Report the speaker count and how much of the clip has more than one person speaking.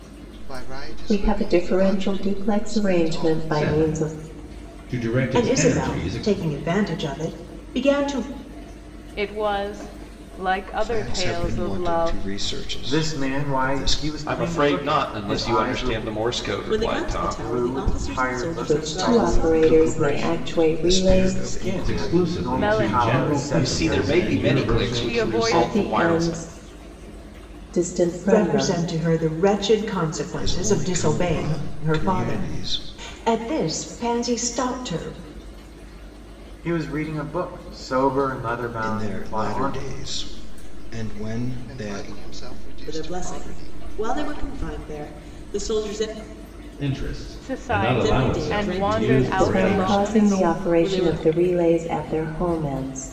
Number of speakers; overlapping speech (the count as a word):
nine, about 53%